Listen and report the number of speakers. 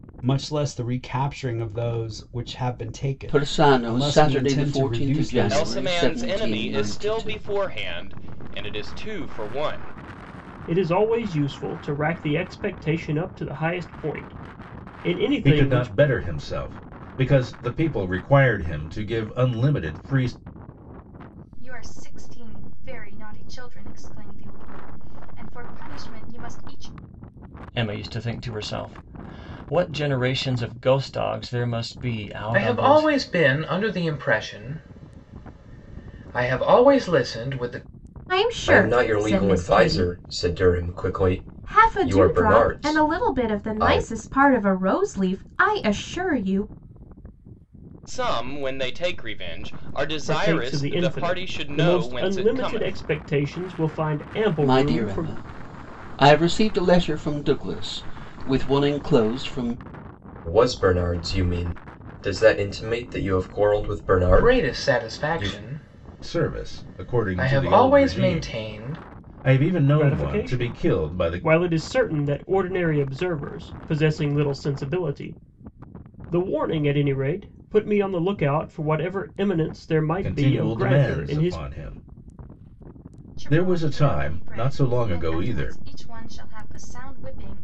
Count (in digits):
10